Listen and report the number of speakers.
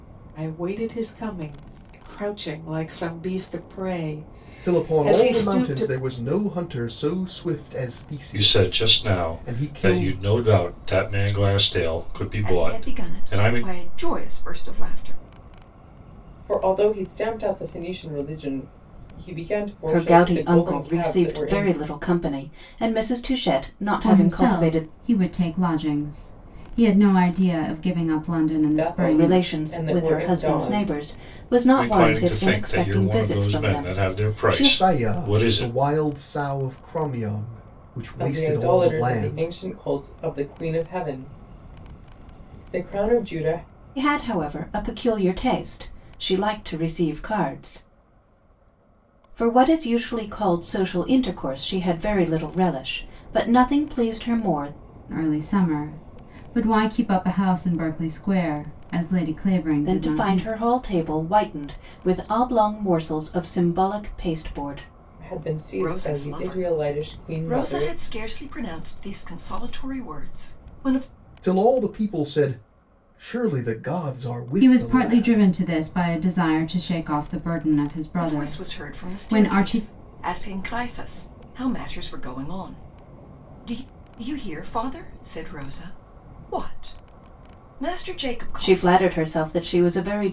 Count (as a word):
seven